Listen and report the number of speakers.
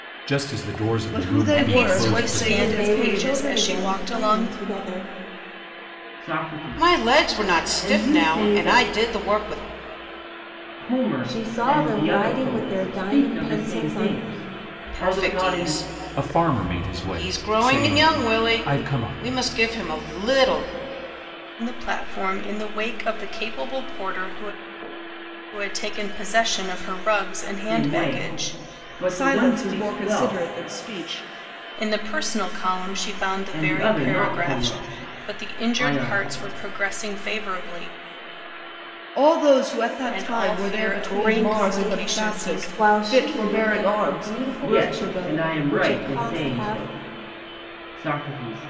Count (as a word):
six